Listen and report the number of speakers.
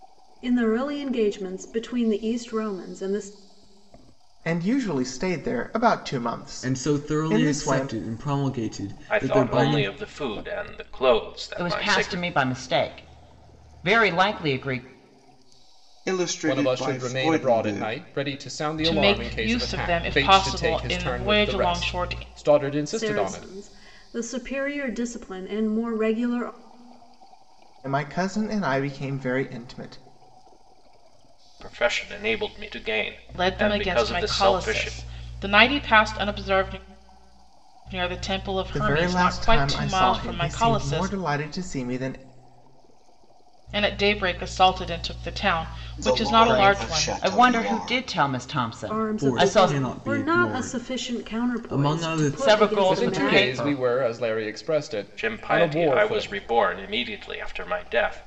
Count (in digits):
8